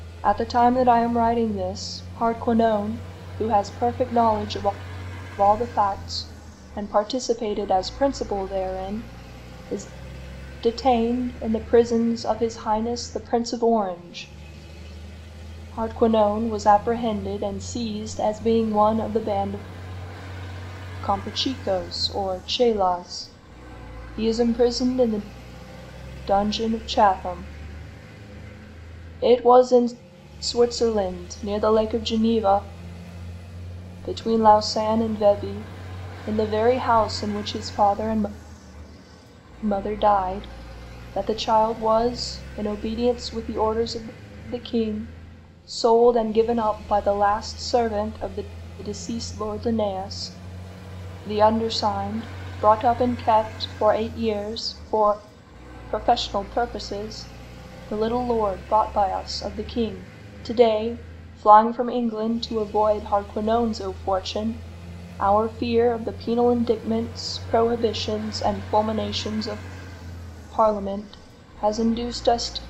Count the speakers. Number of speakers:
1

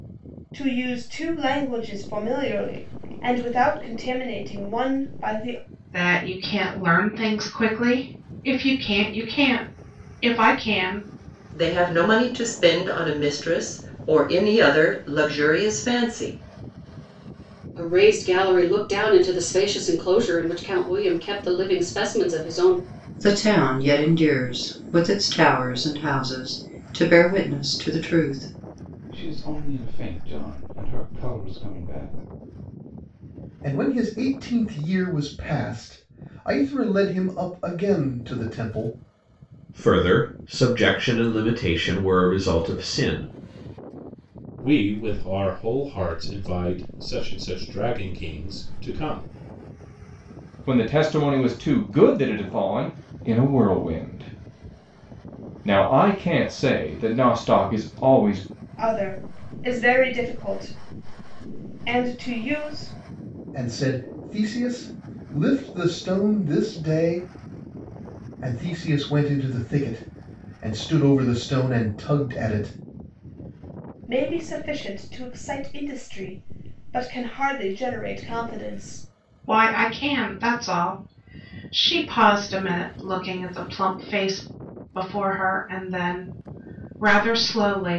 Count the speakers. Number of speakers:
10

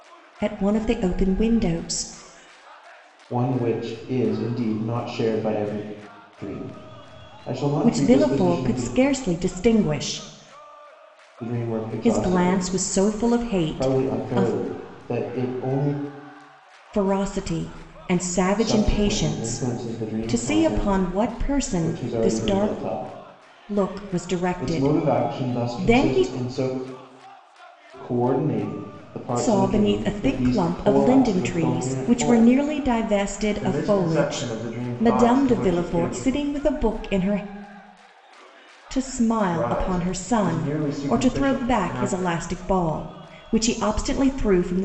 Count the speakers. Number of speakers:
2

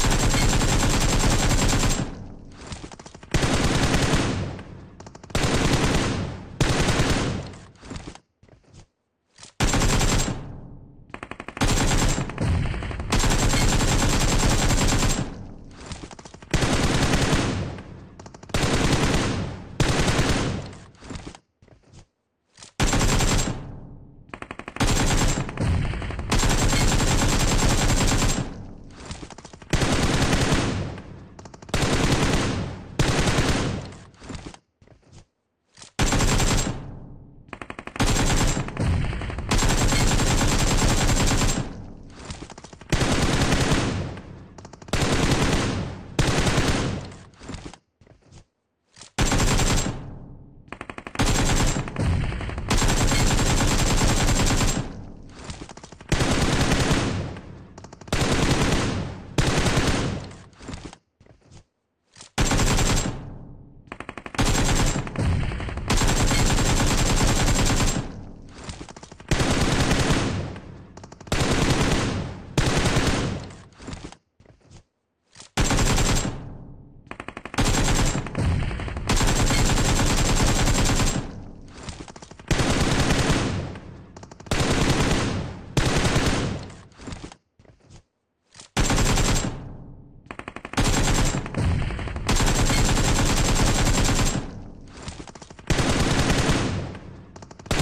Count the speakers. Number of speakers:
0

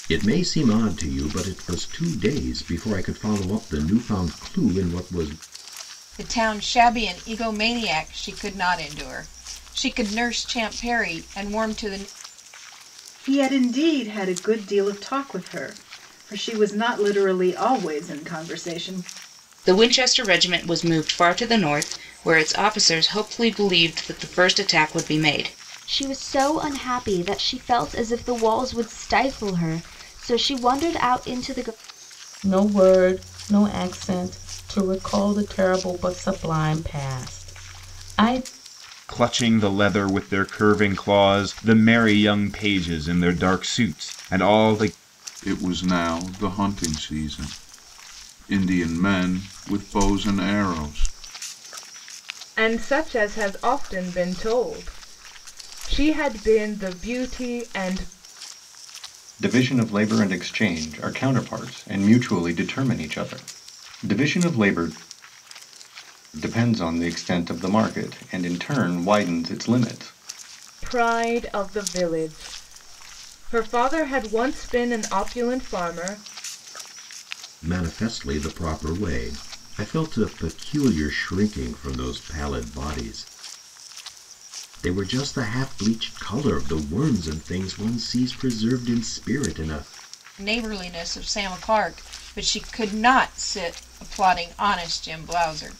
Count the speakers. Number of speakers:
10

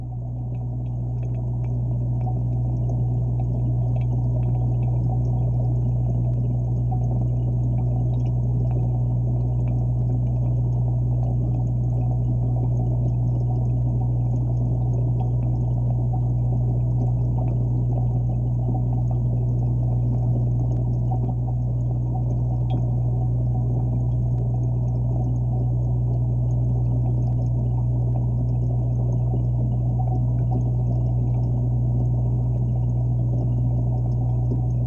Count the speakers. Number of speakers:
0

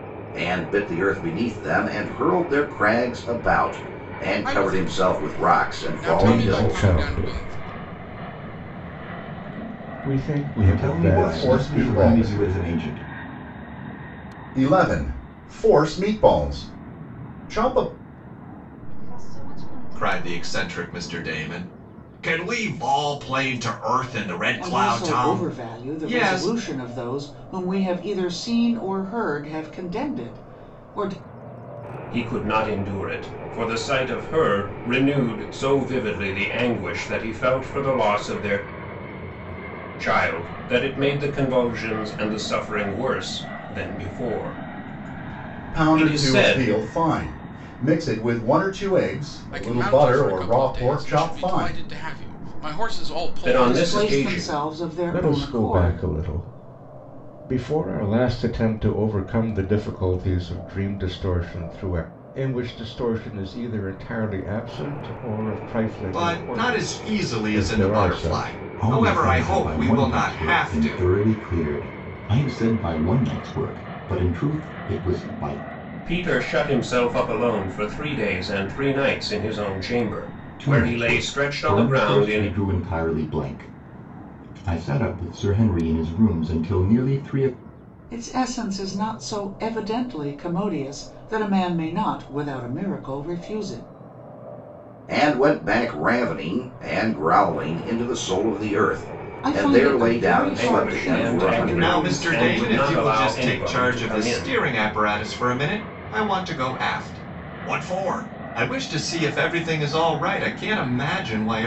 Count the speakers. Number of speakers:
9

